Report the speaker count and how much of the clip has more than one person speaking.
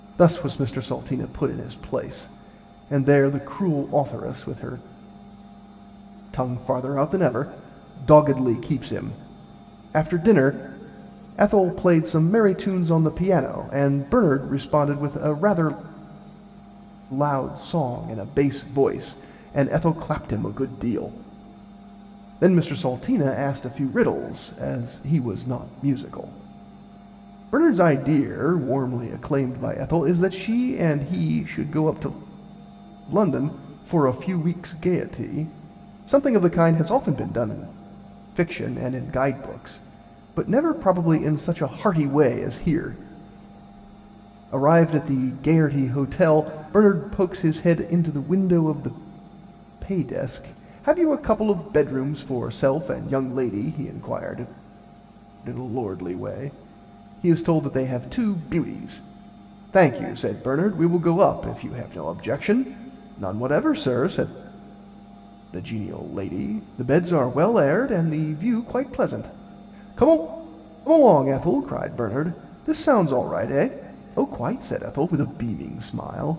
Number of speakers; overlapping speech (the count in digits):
1, no overlap